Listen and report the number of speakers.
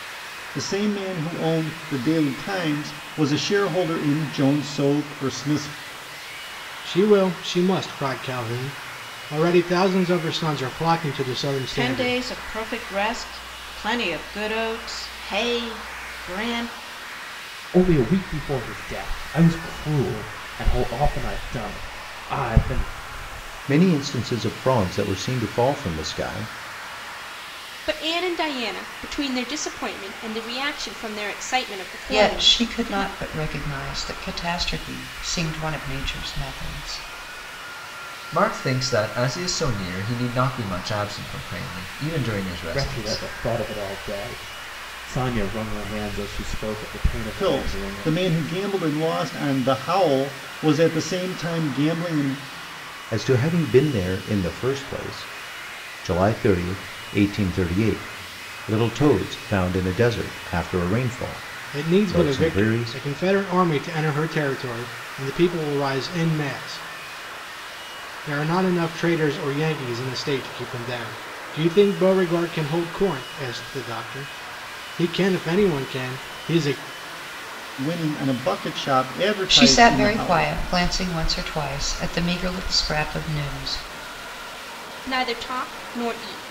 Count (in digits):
8